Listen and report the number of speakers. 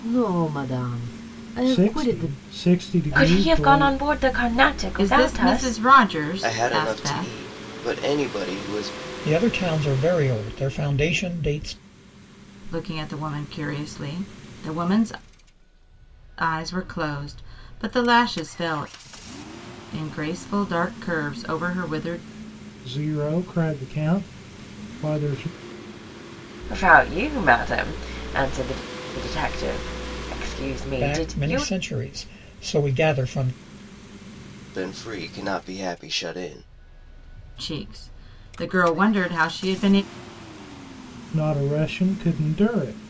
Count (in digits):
6